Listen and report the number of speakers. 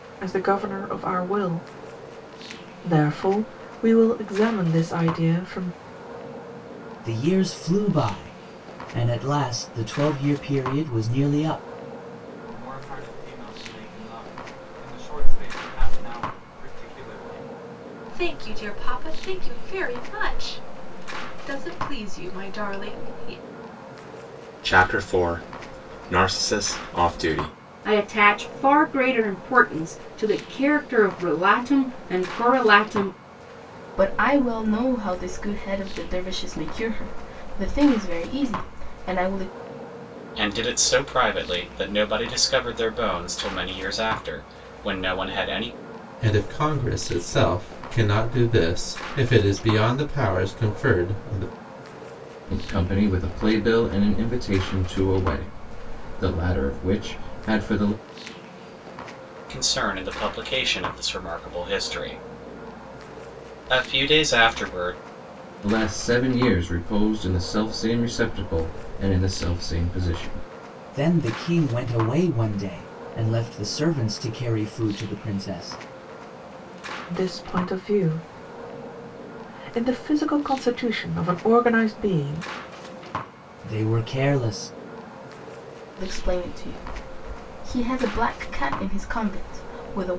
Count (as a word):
ten